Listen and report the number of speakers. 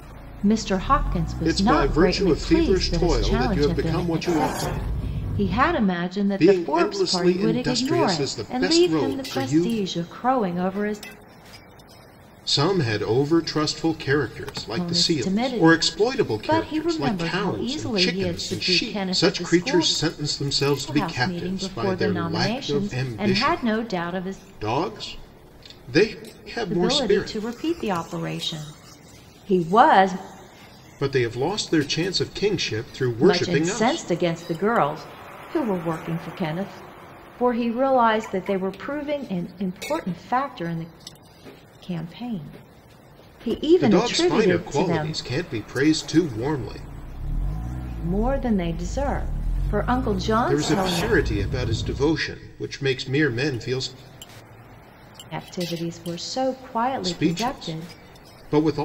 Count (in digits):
2